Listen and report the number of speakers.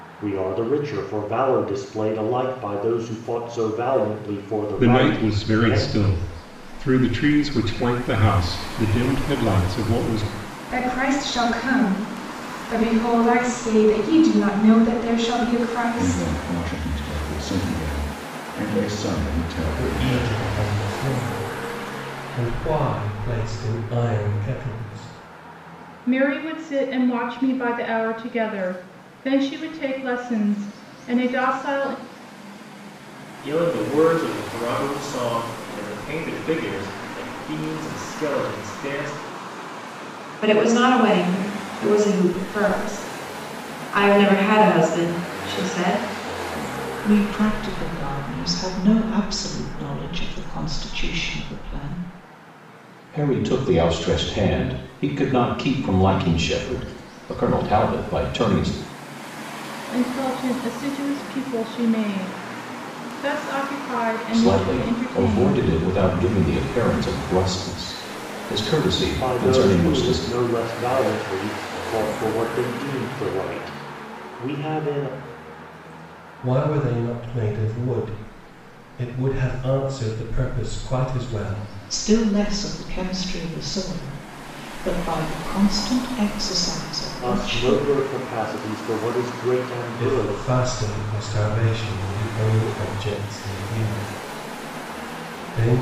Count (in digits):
10